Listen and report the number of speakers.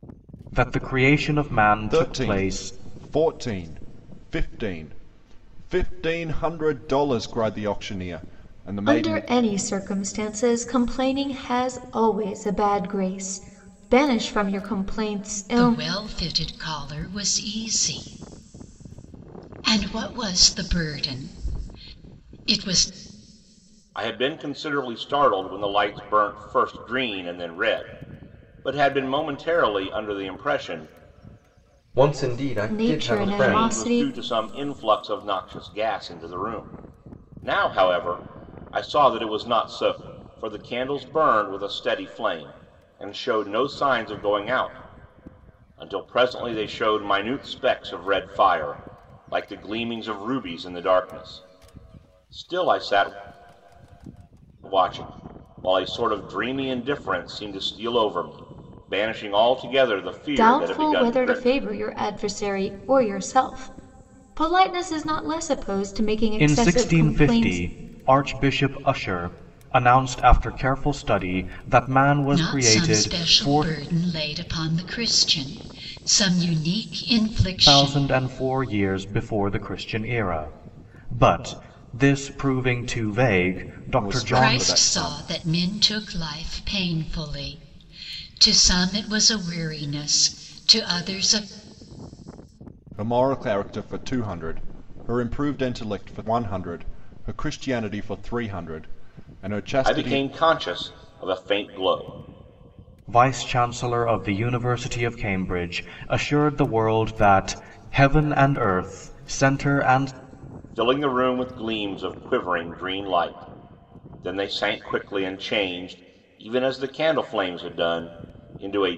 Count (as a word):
six